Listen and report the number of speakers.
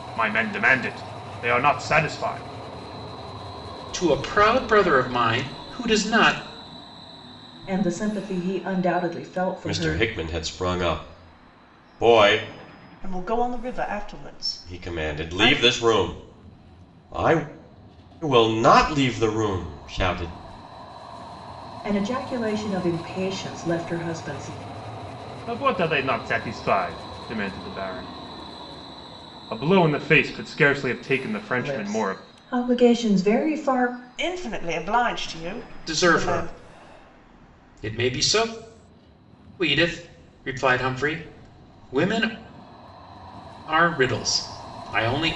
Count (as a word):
five